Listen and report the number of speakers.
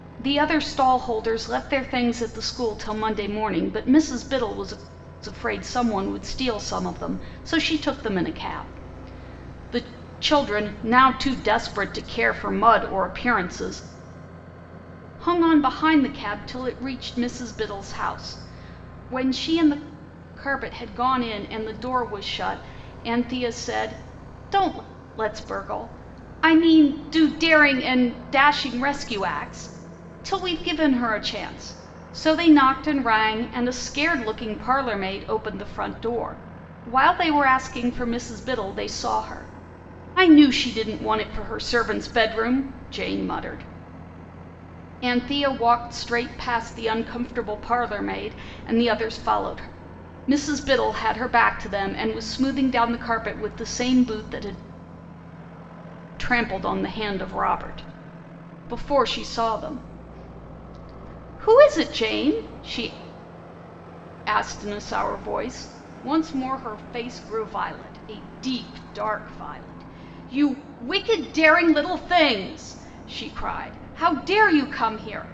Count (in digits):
1